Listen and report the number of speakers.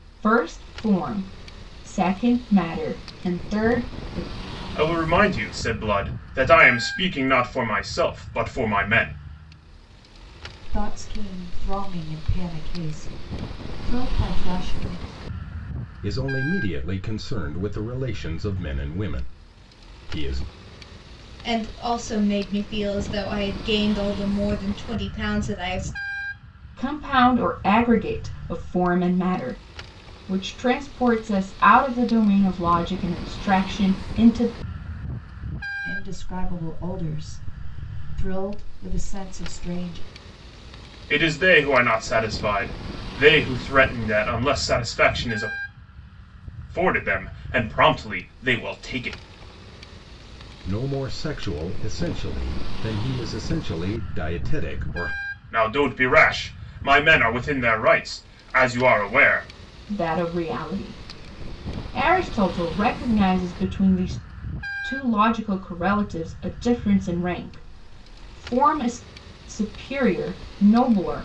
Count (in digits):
5